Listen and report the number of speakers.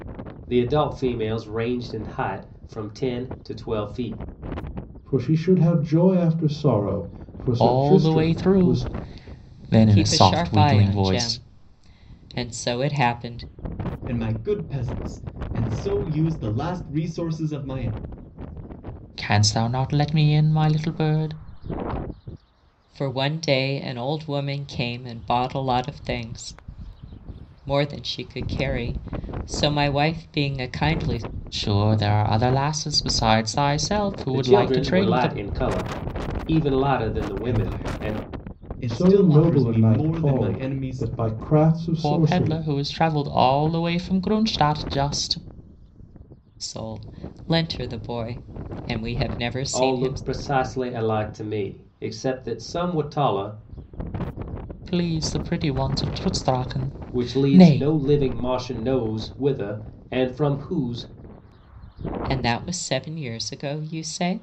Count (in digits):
5